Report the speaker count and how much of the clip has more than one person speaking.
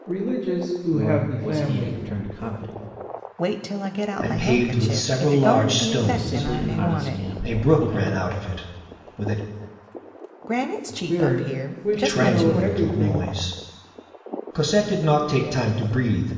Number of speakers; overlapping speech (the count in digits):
4, about 44%